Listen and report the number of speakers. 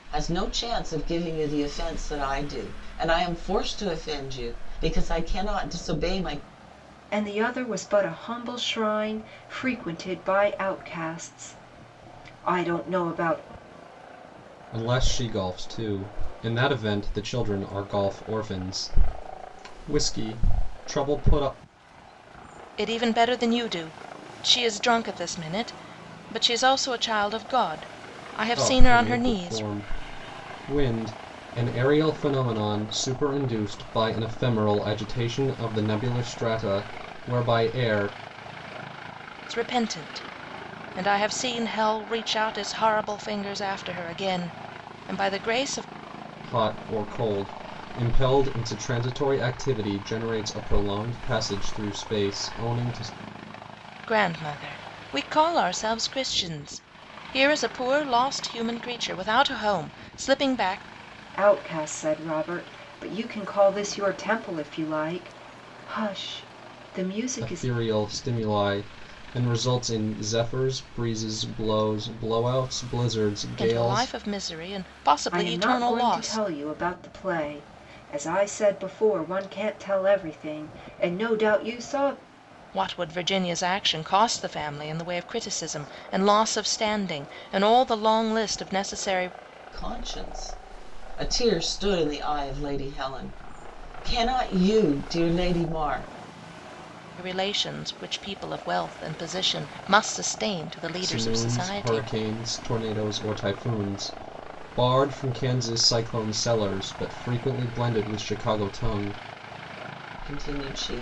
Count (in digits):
4